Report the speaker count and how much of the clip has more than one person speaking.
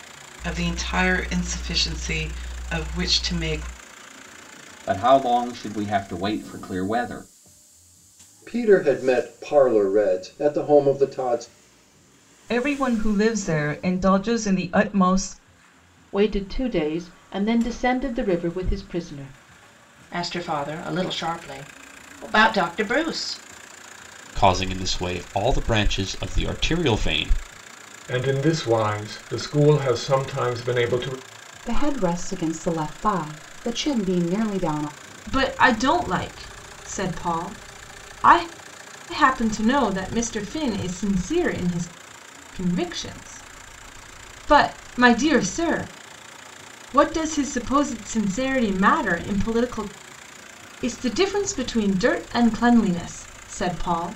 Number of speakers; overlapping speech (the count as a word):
ten, no overlap